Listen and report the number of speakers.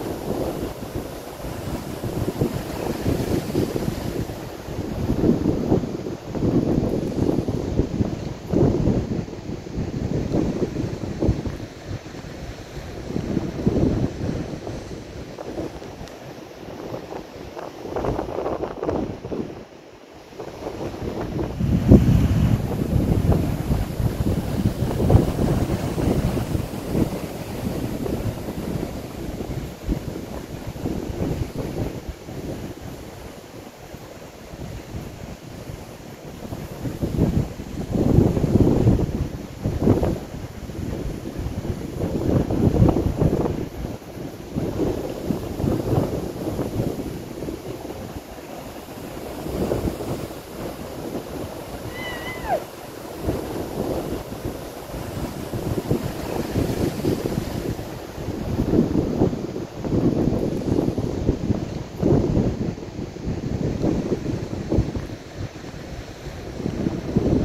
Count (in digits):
0